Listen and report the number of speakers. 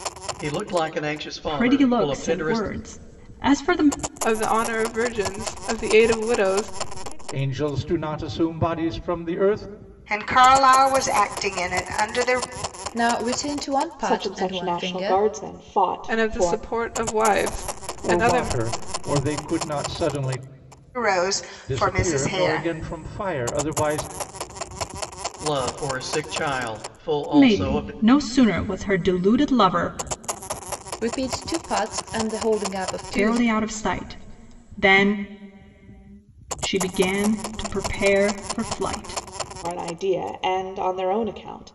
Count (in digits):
7